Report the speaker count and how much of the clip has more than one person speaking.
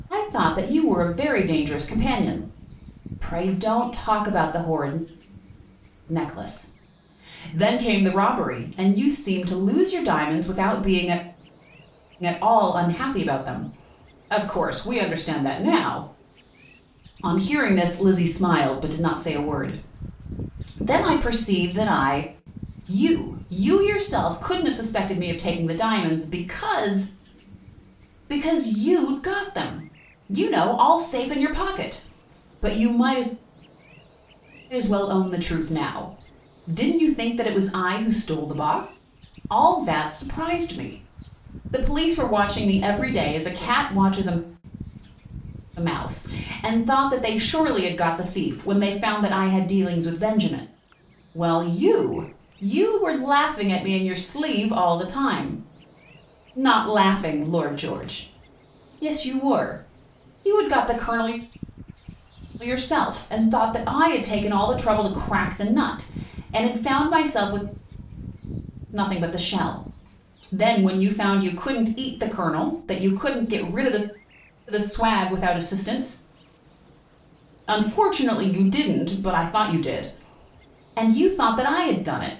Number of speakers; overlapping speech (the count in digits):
1, no overlap